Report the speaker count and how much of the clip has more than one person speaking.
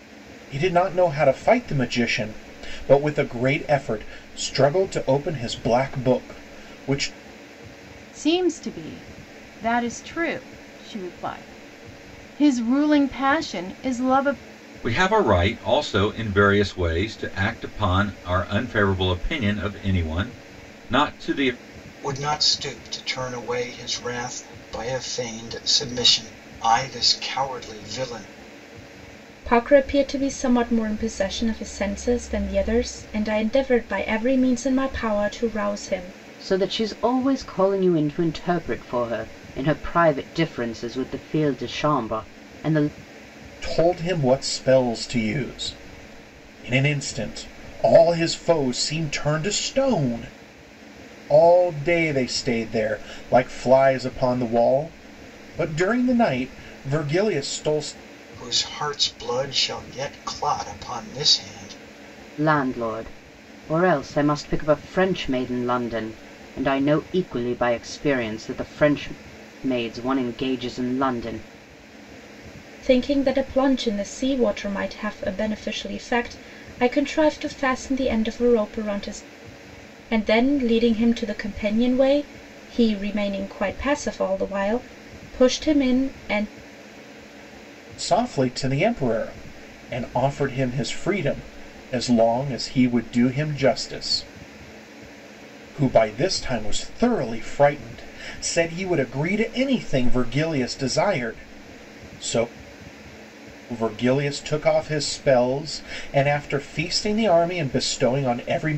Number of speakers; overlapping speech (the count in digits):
6, no overlap